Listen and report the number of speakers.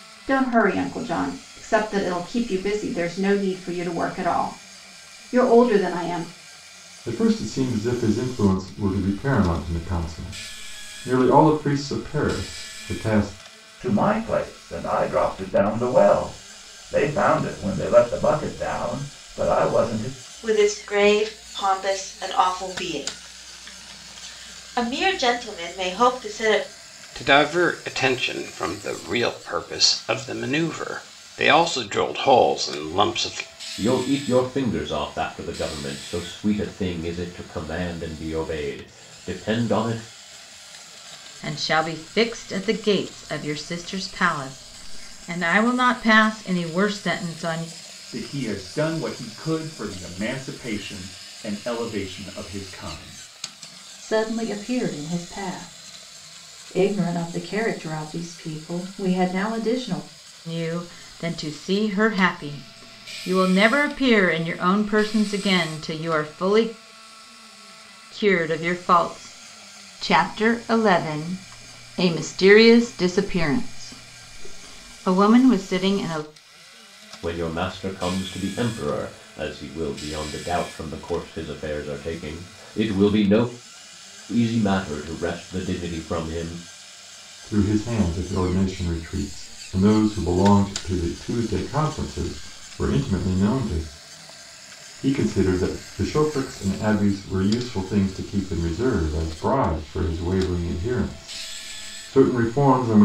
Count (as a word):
nine